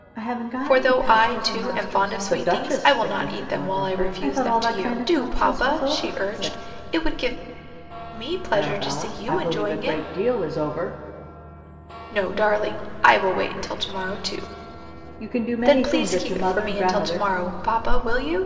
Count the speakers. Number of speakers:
two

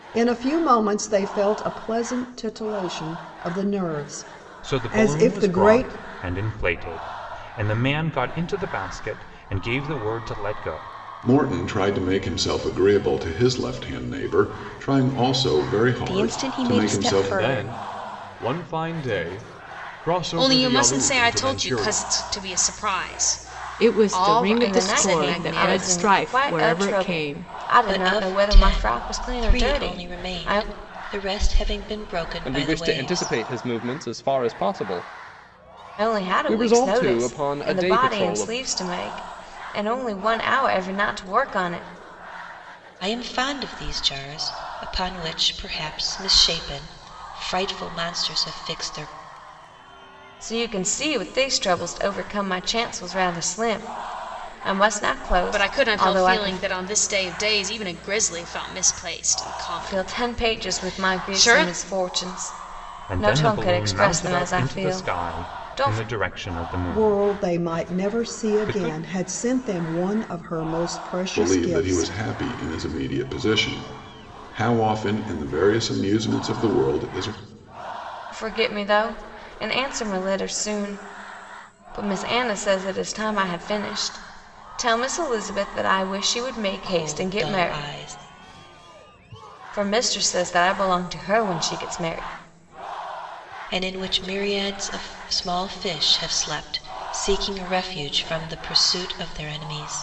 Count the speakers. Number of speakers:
ten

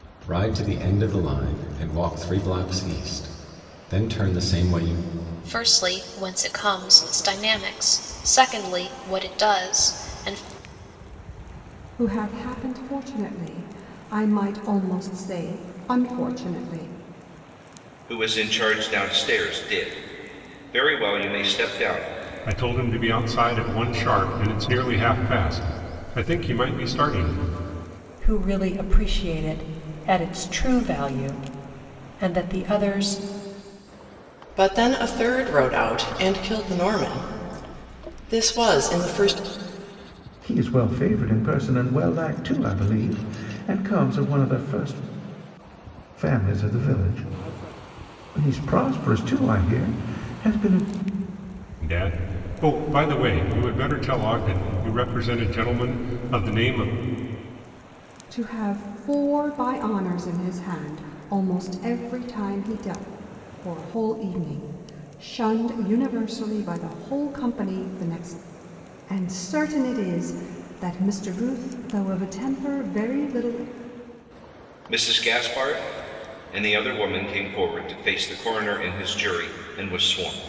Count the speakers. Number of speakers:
eight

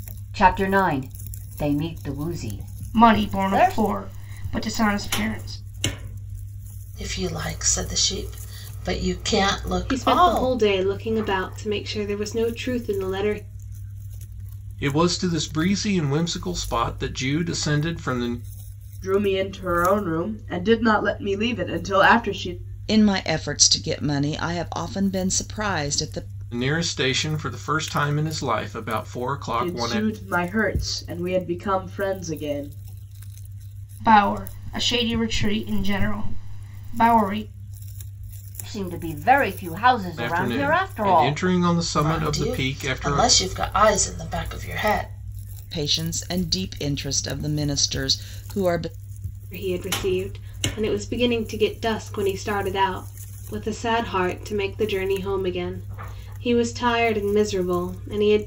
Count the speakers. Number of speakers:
seven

